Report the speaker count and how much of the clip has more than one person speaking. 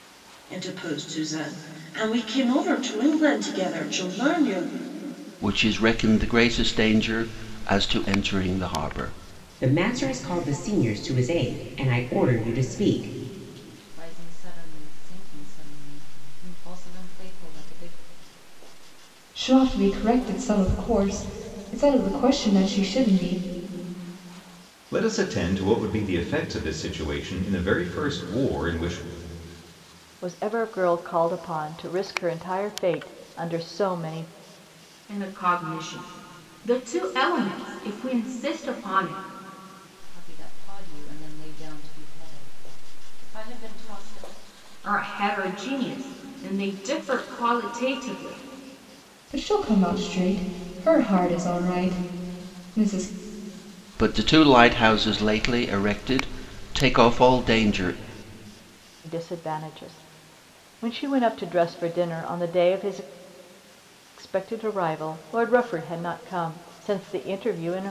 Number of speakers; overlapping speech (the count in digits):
8, no overlap